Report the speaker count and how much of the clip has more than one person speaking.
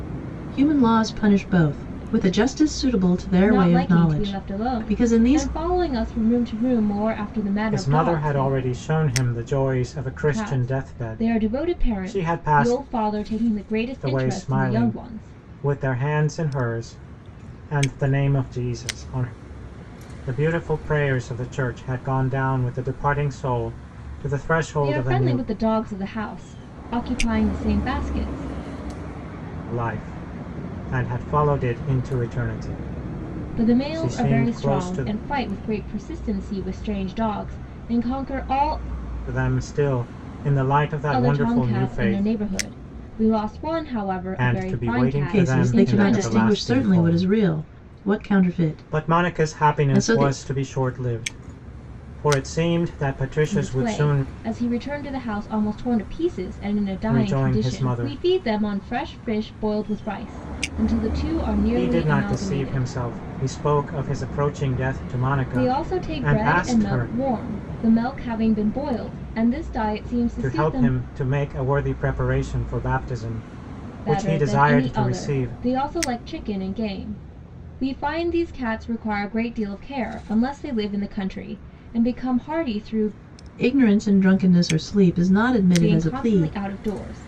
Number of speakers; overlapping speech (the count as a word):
three, about 26%